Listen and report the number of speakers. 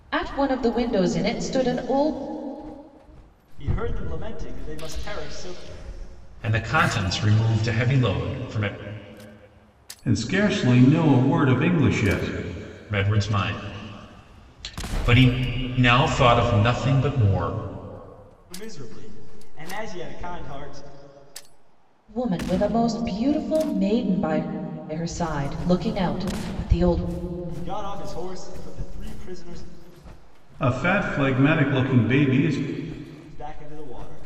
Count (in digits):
4